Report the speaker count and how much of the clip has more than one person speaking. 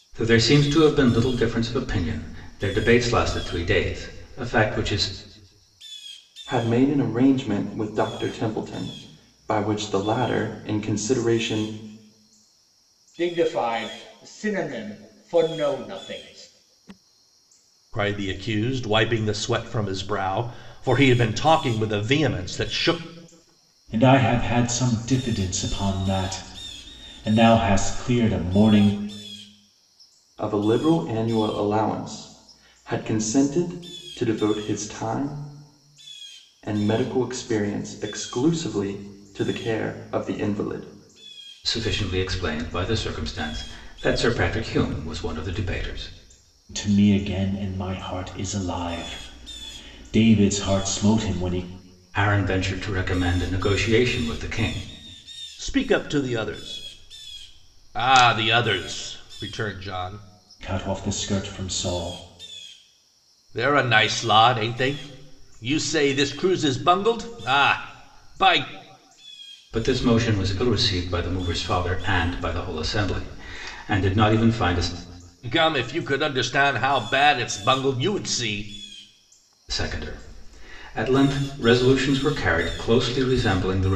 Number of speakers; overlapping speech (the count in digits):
5, no overlap